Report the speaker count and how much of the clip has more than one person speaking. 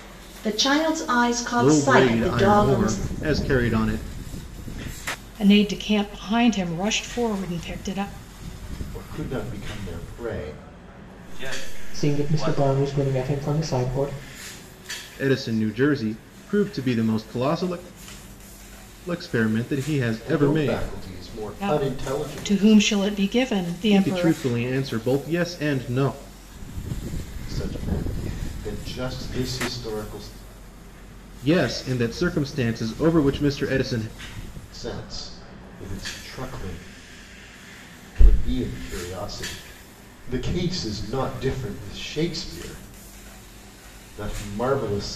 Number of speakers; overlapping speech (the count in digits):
6, about 10%